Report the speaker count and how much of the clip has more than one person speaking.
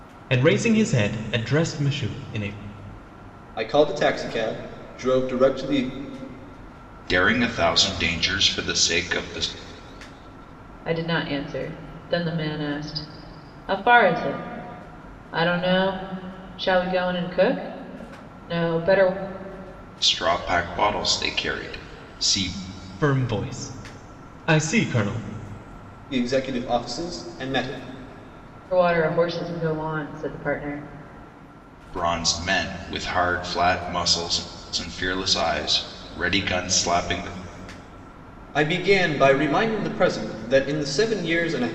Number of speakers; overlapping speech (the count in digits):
4, no overlap